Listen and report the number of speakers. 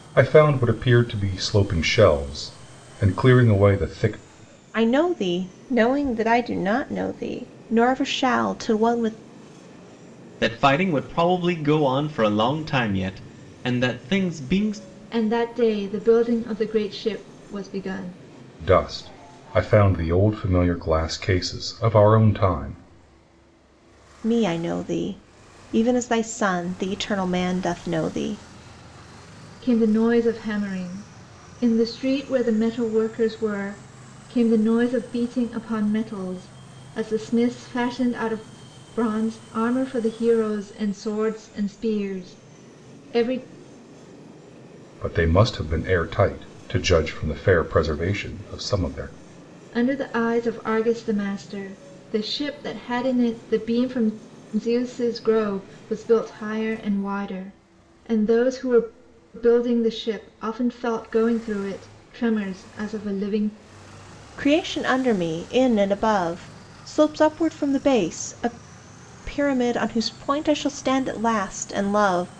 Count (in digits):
4